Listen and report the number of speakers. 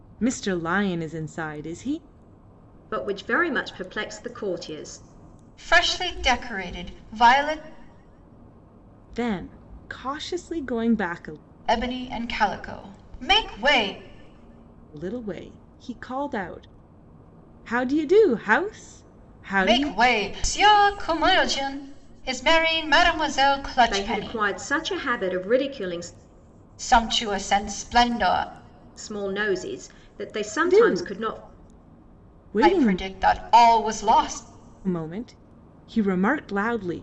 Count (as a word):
three